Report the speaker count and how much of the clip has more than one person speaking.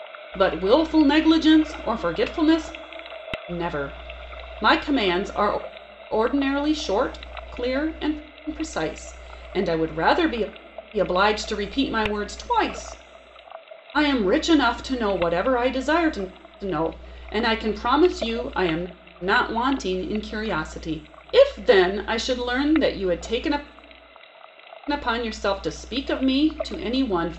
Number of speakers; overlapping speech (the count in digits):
1, no overlap